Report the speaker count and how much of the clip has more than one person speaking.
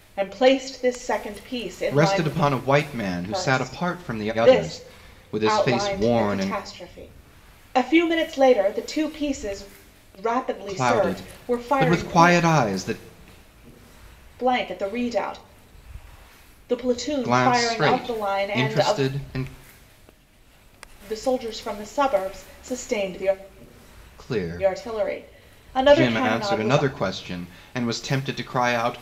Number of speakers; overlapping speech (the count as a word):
two, about 32%